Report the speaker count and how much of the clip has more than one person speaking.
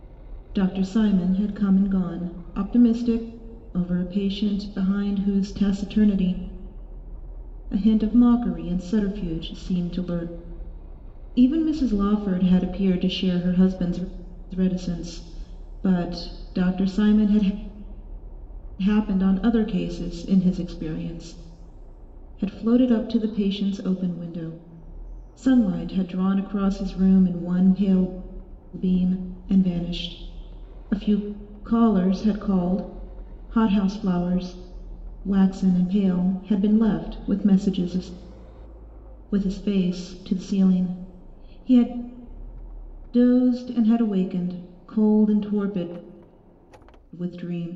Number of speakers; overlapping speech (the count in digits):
1, no overlap